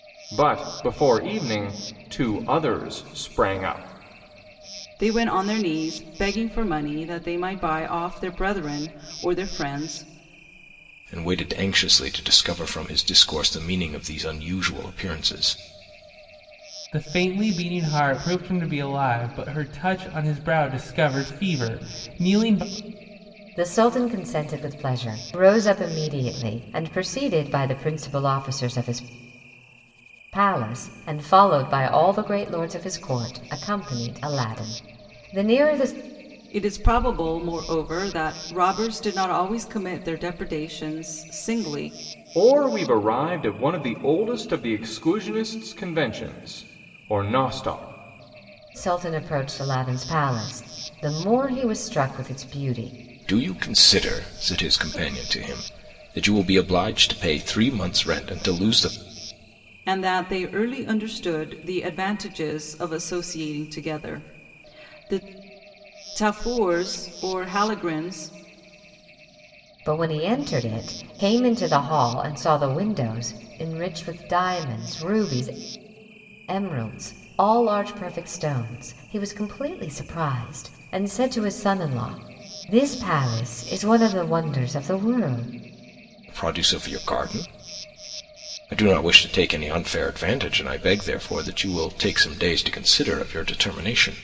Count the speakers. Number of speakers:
5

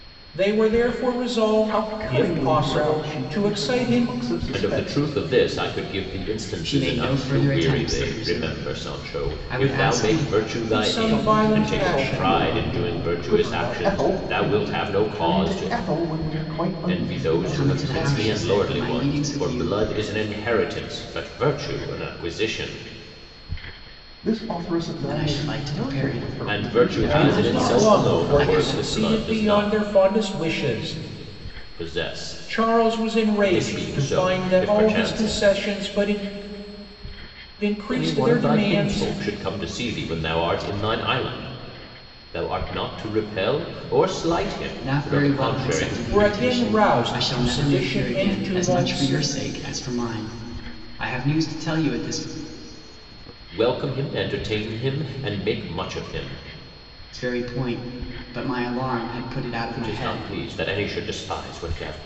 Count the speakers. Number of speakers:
4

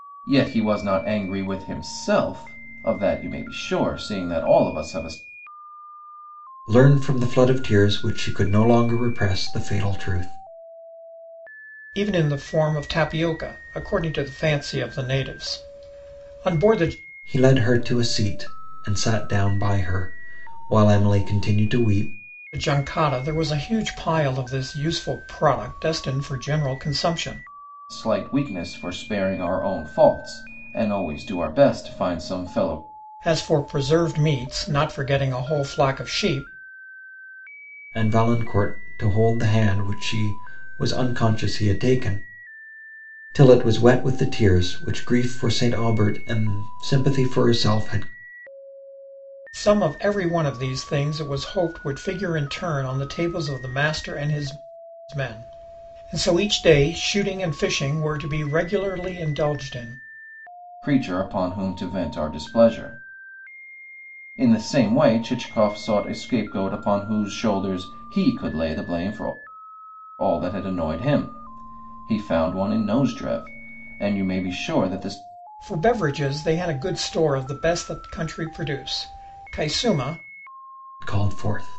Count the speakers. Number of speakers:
3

